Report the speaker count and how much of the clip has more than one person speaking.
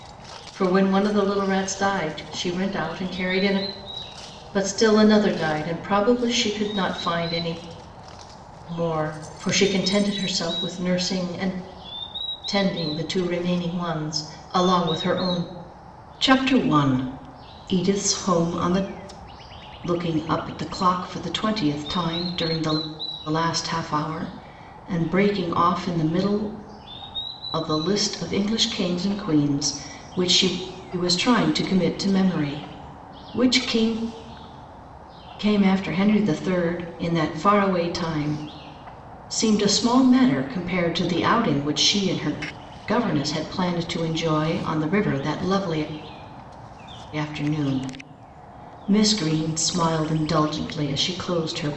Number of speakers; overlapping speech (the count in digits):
1, no overlap